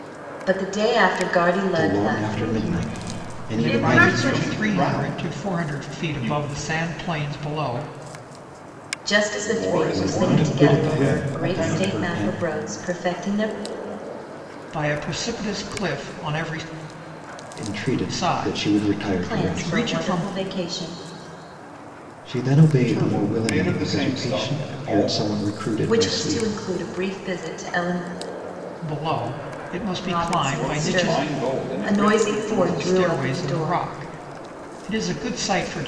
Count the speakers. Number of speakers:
5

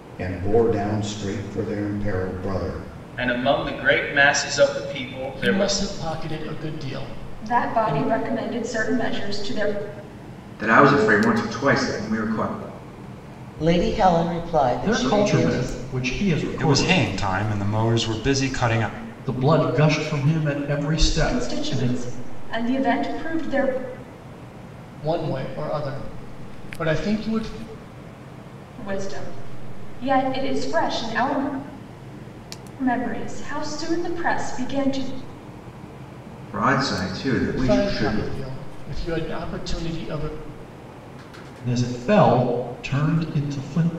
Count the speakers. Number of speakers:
8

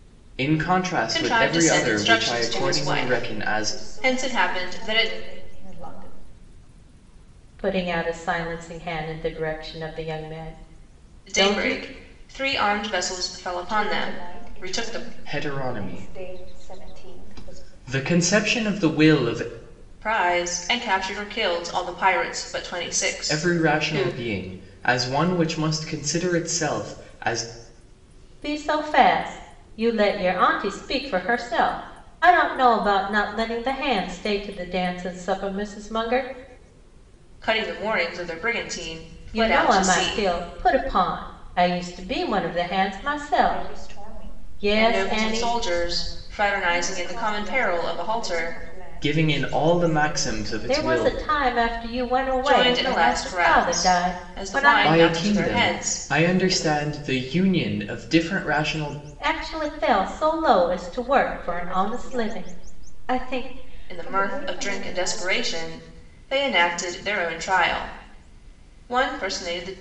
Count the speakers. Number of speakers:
4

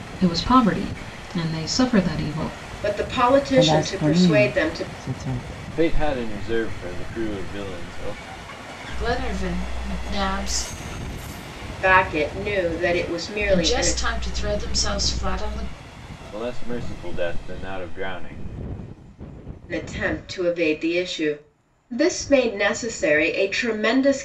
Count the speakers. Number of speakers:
5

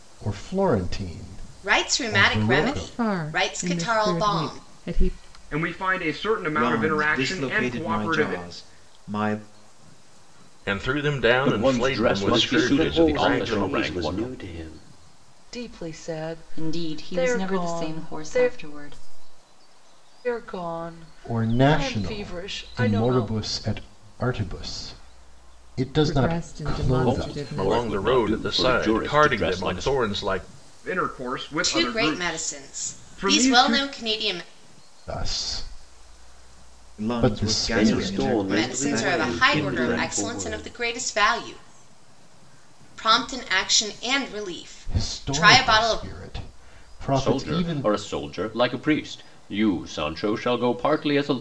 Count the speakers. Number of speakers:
10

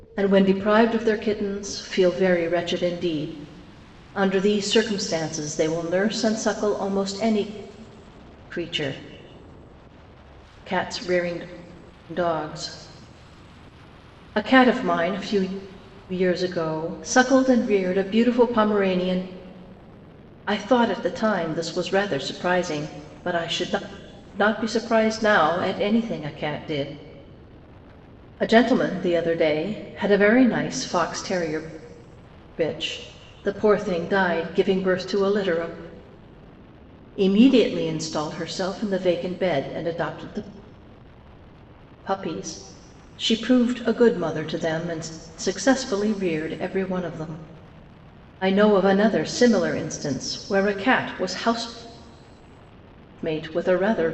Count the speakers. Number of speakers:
1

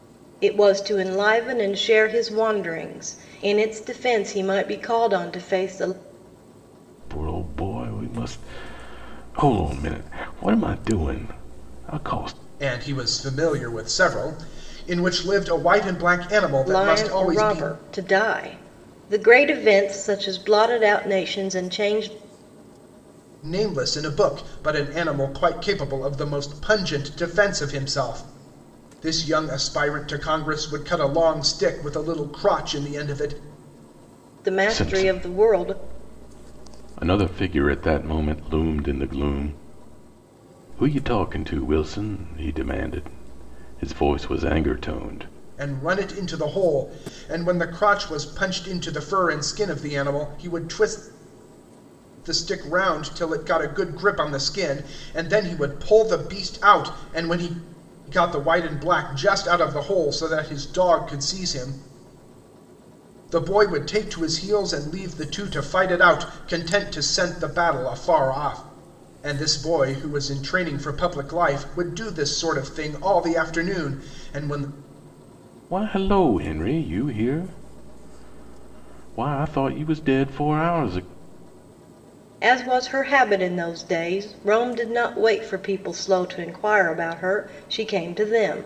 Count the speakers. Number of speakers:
3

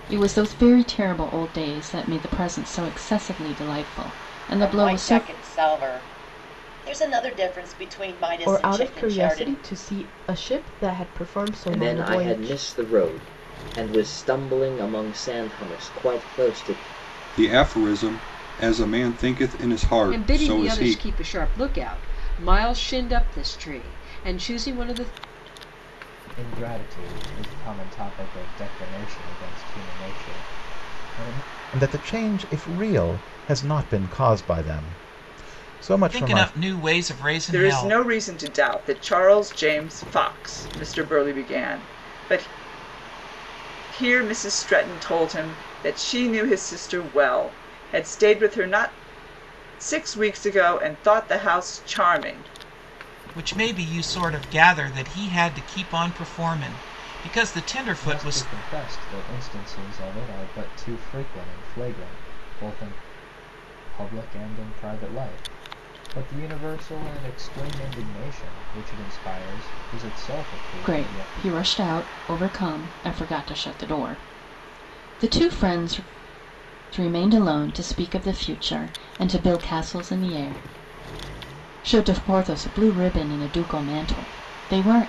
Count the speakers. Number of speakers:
10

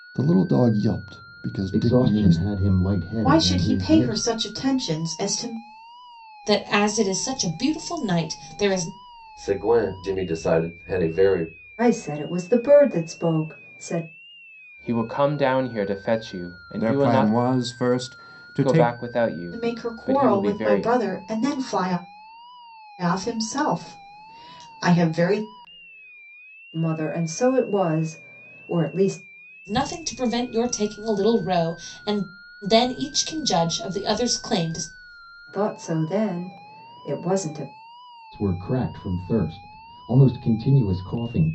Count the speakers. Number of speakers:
8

